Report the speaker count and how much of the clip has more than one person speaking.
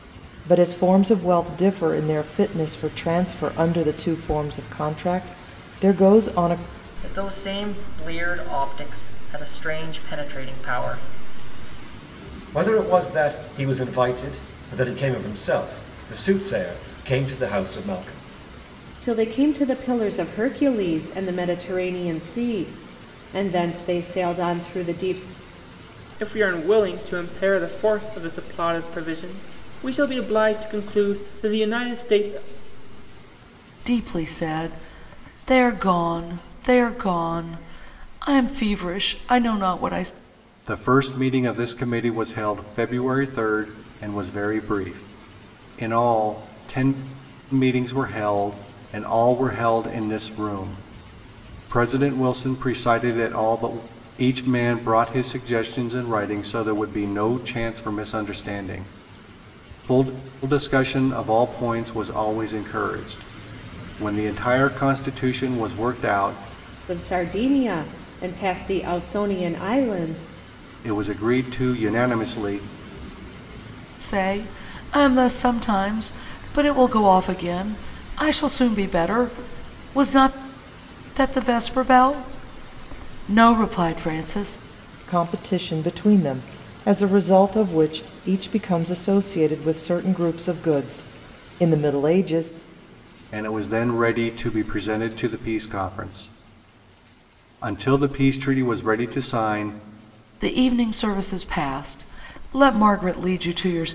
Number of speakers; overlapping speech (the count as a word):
seven, no overlap